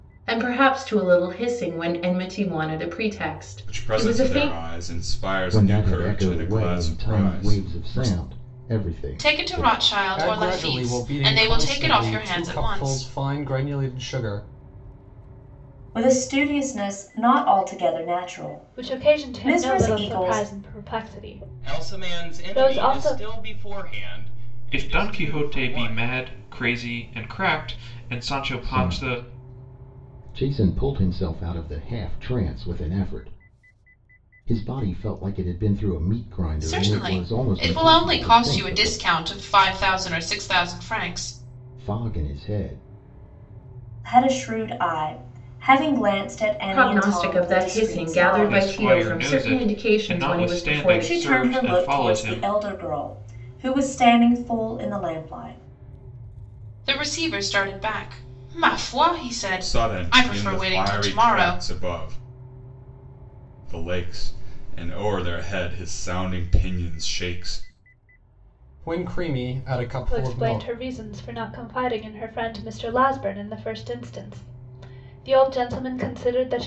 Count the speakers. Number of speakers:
9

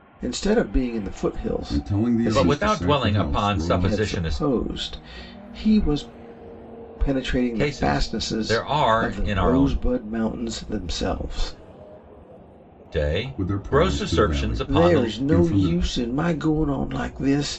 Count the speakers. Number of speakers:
3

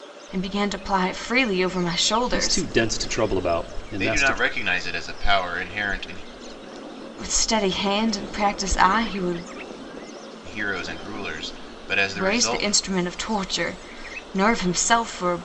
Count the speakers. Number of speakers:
3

